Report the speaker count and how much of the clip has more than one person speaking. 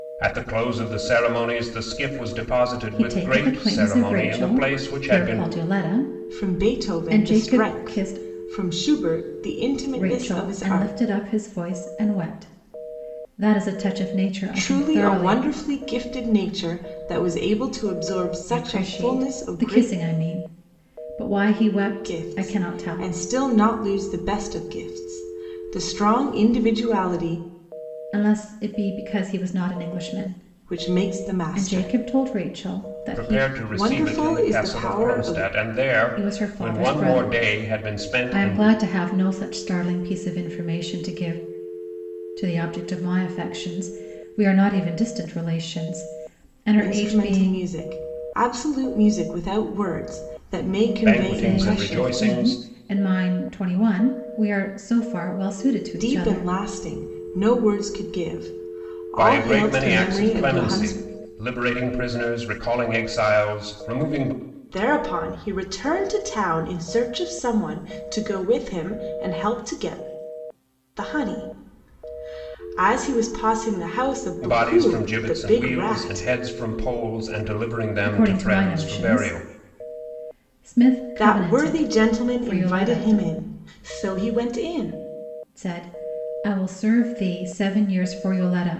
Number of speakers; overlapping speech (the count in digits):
3, about 30%